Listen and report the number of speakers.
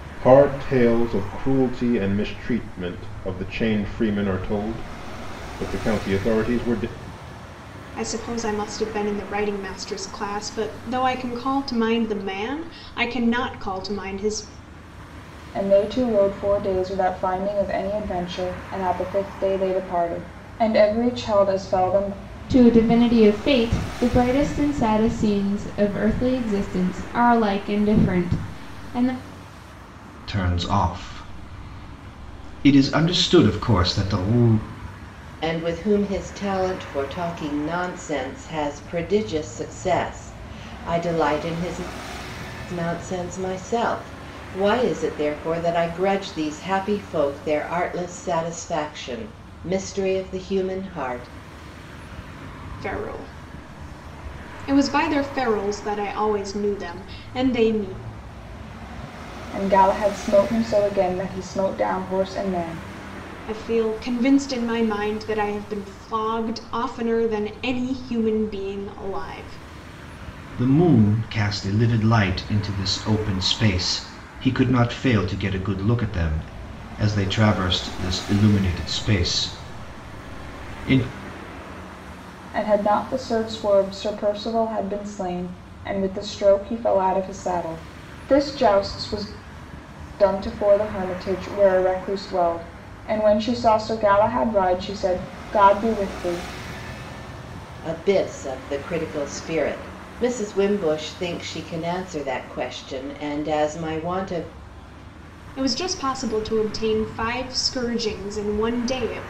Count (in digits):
6